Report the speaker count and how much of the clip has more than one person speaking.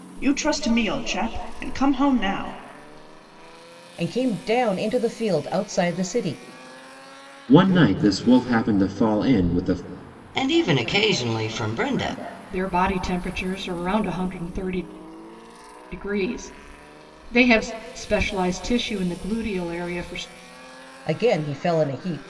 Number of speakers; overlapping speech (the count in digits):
5, no overlap